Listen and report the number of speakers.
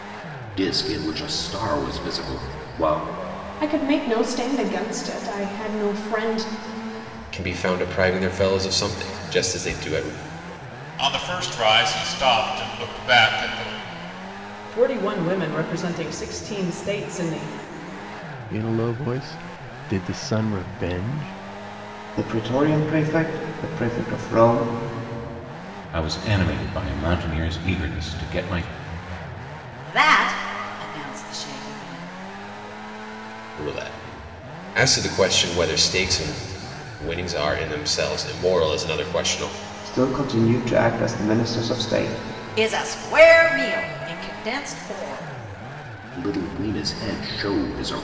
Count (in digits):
9